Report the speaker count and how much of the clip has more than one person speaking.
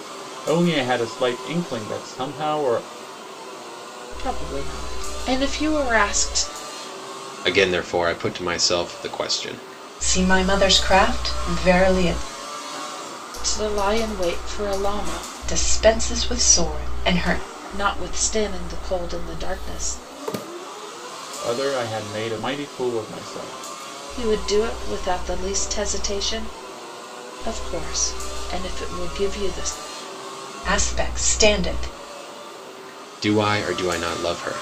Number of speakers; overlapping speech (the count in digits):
4, no overlap